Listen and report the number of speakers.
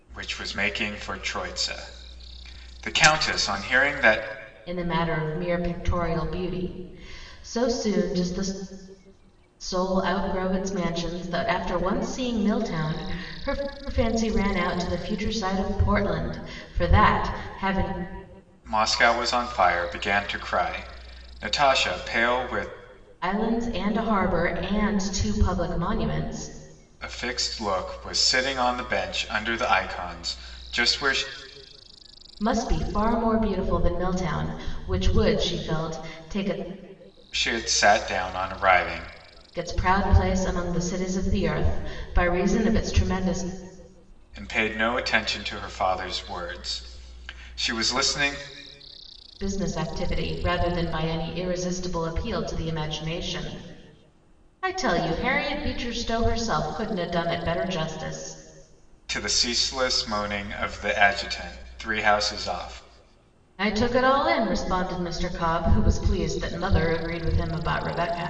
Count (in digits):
2